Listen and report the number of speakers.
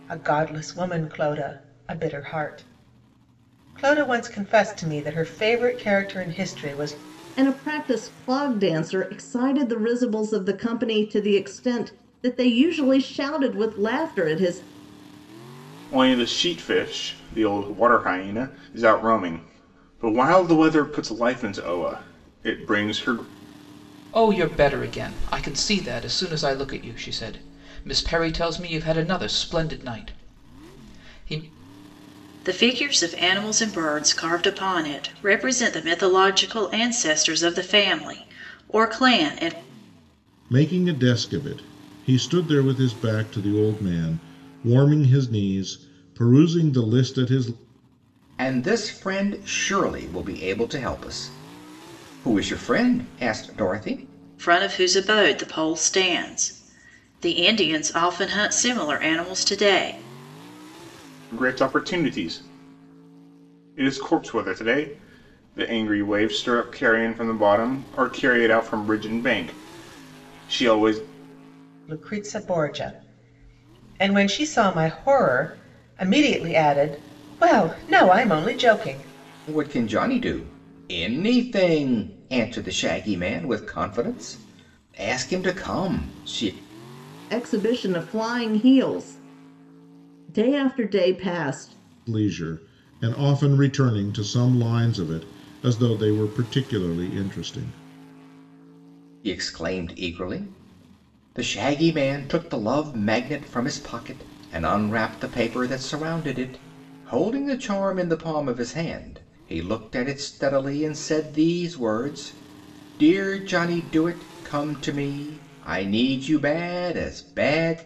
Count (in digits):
7